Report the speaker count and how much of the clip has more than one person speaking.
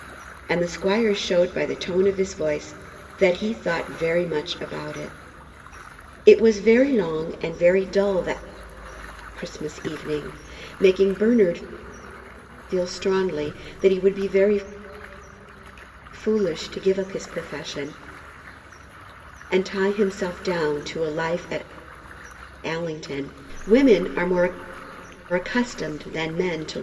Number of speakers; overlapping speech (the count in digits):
1, no overlap